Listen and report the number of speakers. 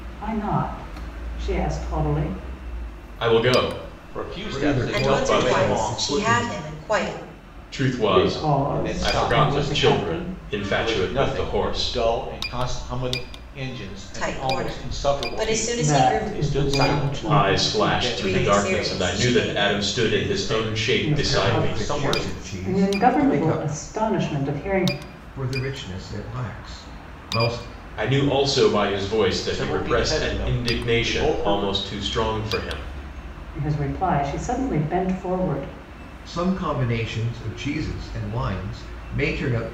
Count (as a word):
five